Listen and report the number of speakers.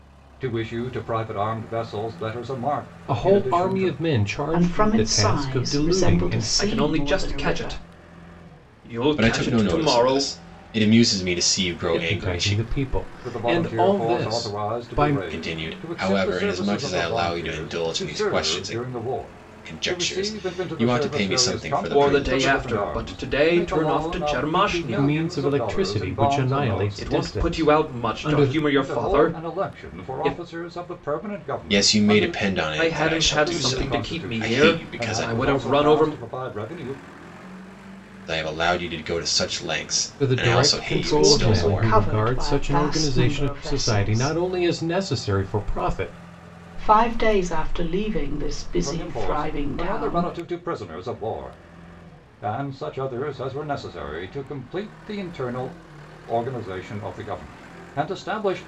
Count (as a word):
five